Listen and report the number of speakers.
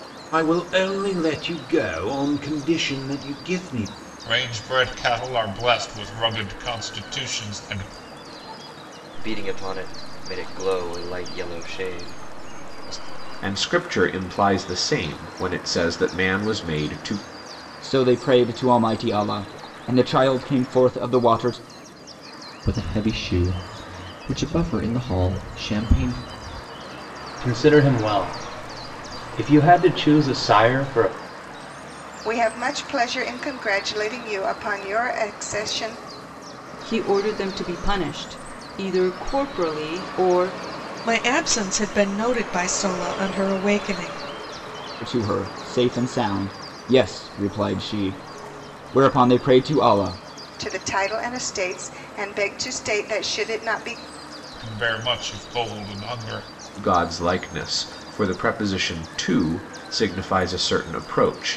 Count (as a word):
ten